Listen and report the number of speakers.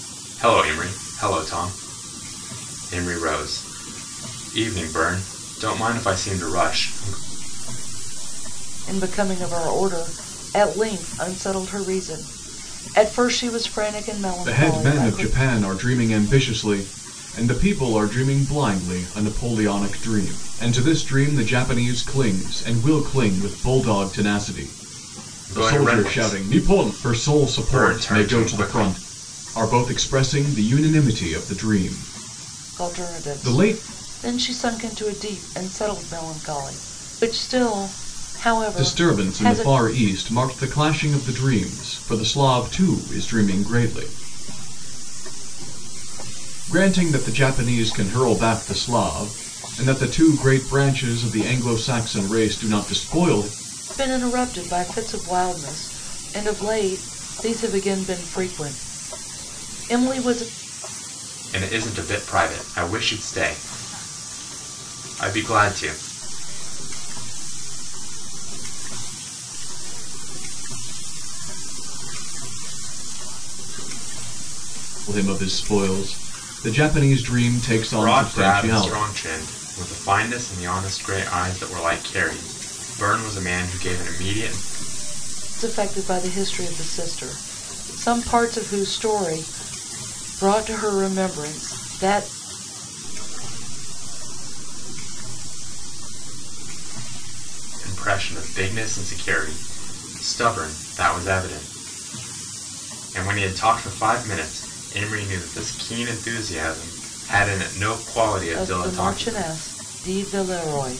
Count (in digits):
4